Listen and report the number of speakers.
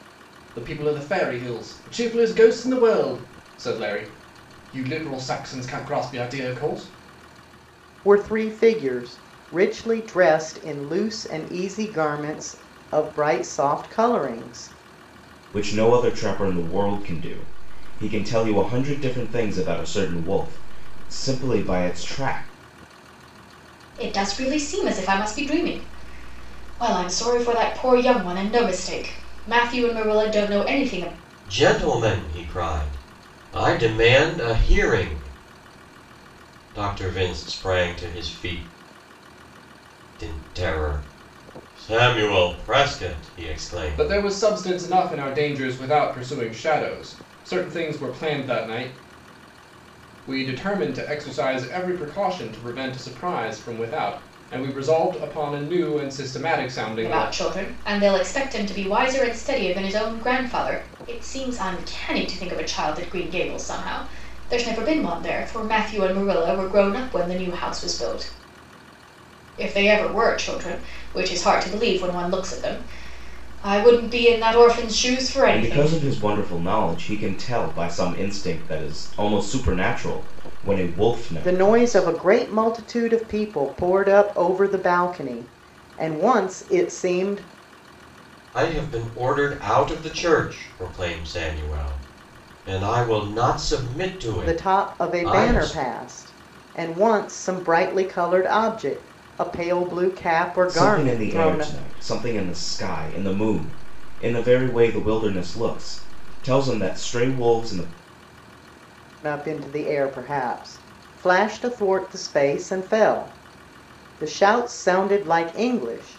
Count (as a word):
five